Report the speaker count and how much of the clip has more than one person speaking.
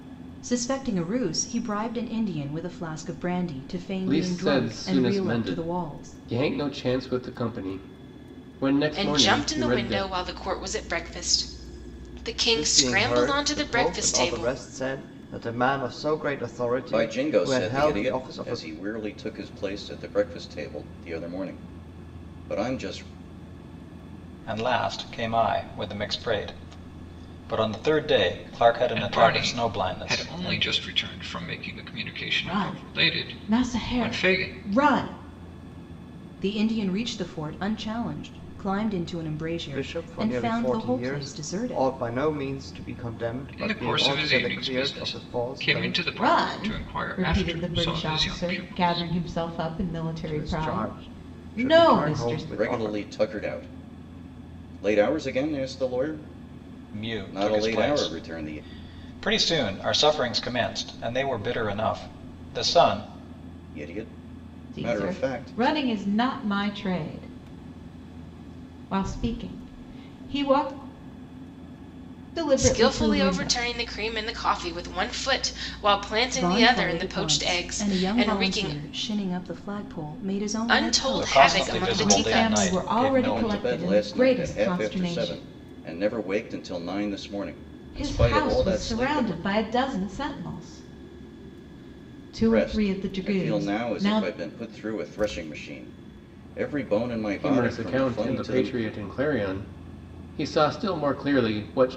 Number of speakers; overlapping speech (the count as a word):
eight, about 37%